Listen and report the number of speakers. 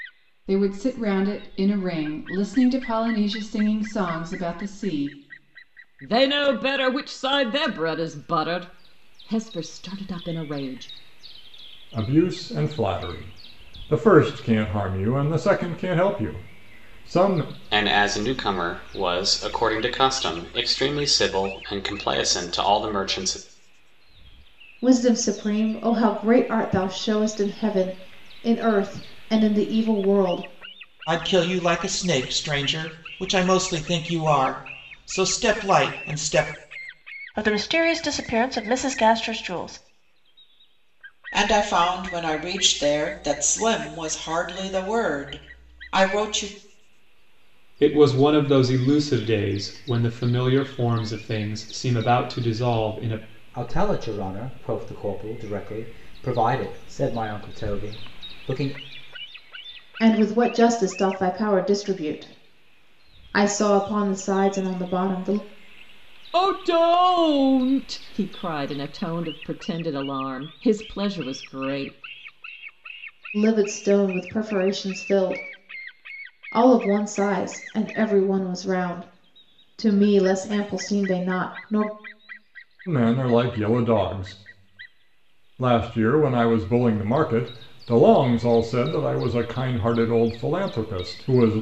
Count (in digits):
10